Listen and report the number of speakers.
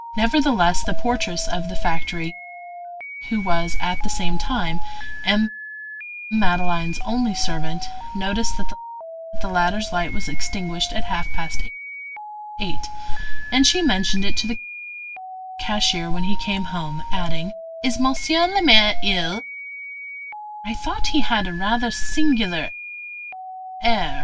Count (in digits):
1